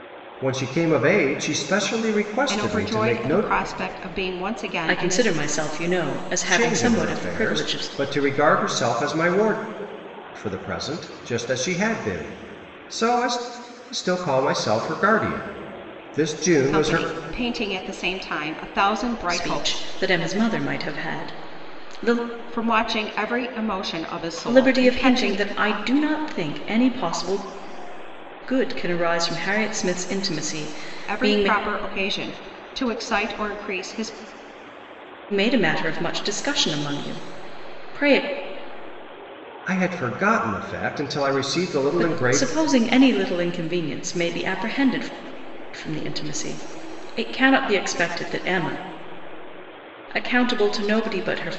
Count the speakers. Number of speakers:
three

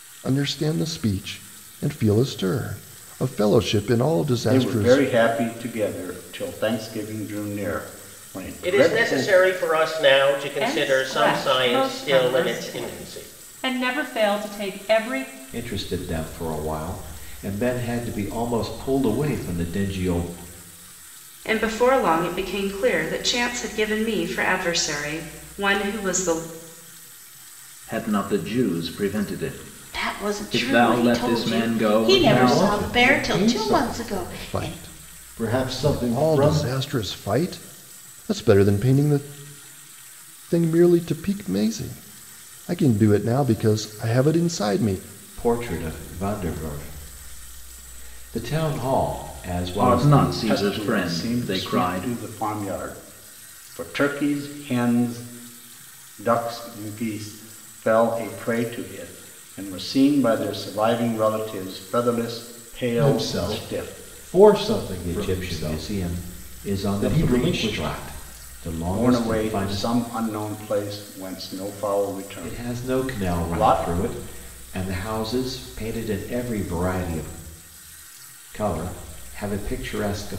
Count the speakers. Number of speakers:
nine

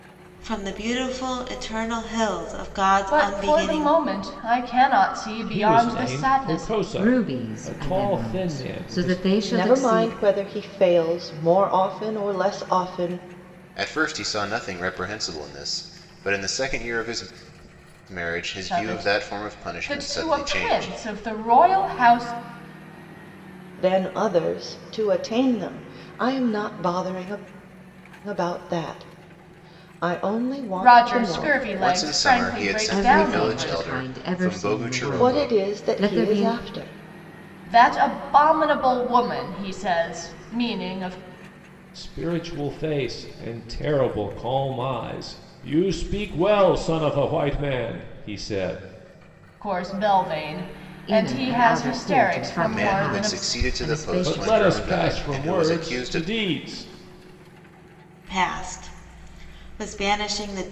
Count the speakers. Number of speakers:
six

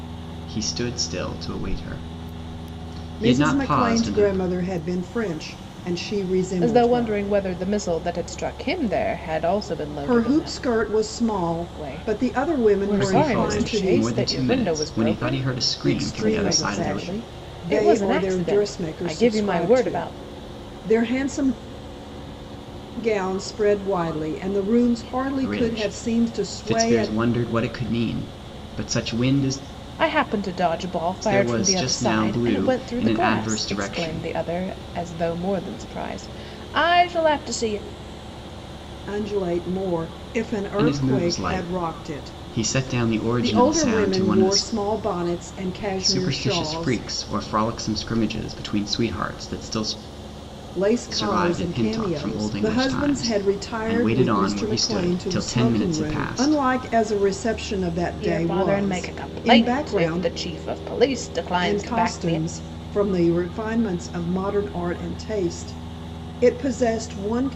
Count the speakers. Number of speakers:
three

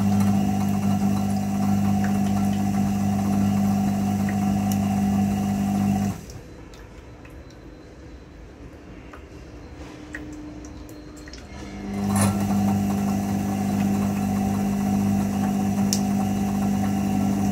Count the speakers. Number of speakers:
zero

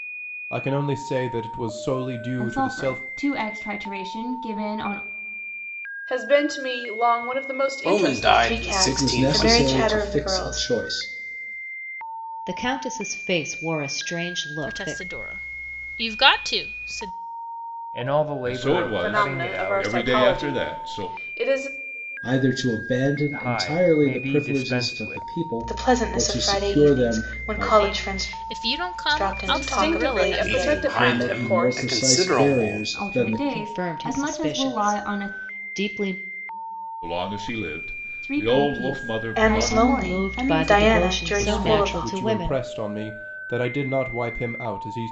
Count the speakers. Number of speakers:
ten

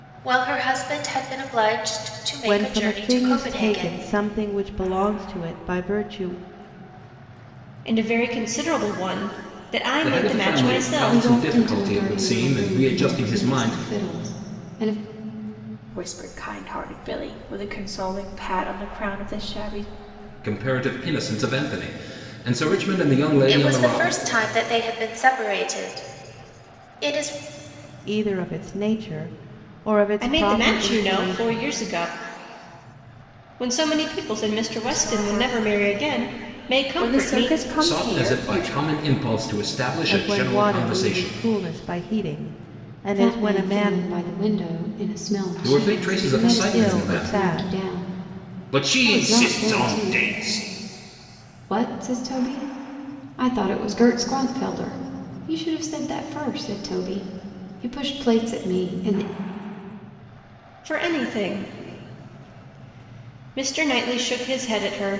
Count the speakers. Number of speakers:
six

